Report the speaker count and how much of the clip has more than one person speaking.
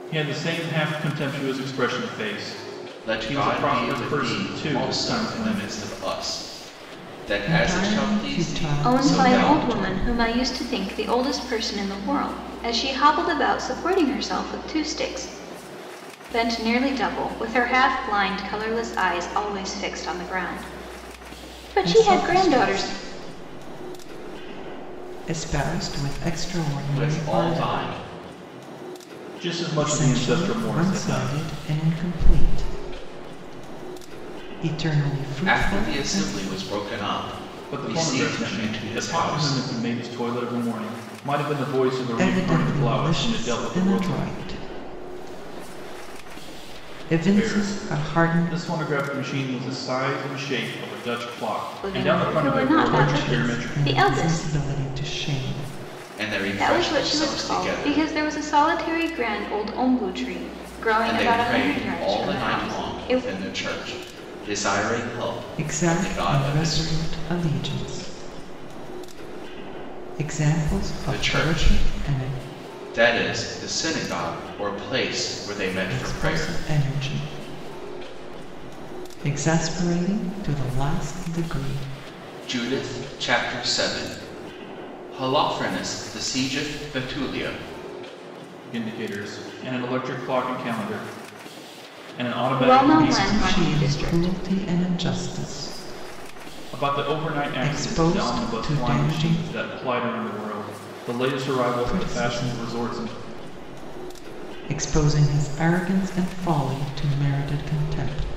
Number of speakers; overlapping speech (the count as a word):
four, about 29%